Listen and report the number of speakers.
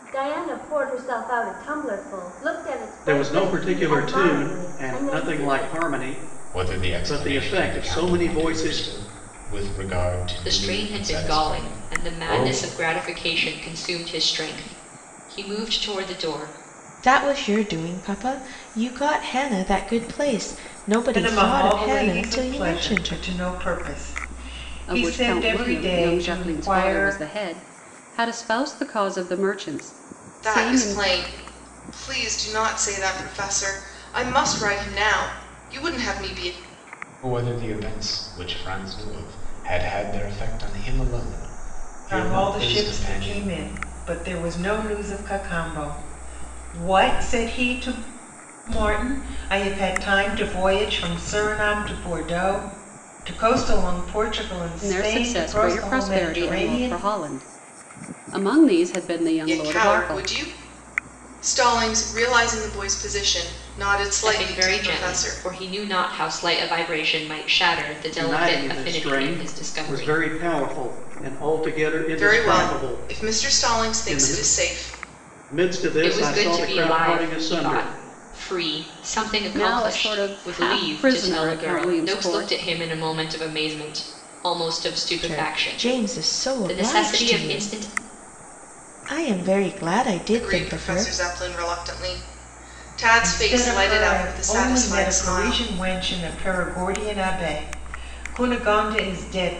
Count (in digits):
8